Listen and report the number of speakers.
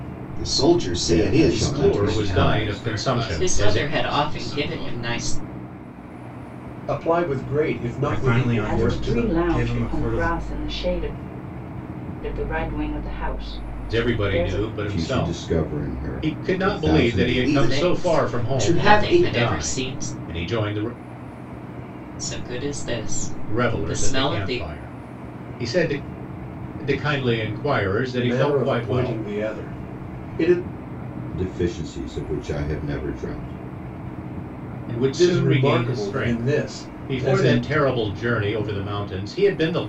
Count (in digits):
8